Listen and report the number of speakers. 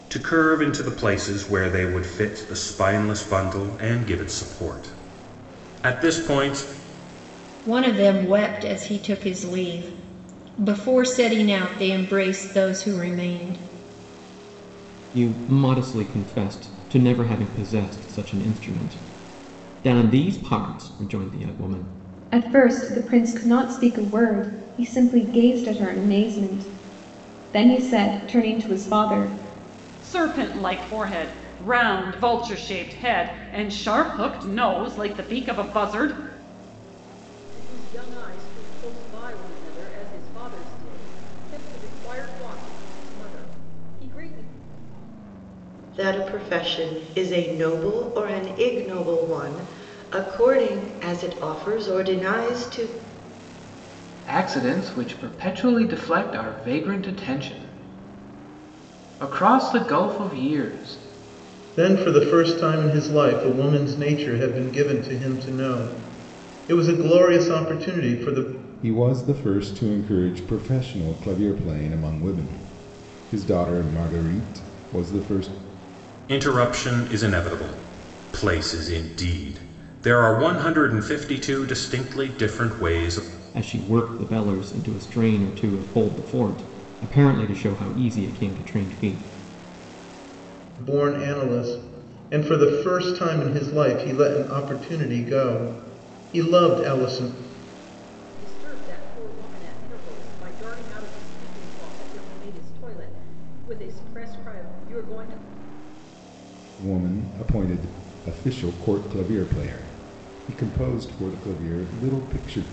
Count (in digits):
10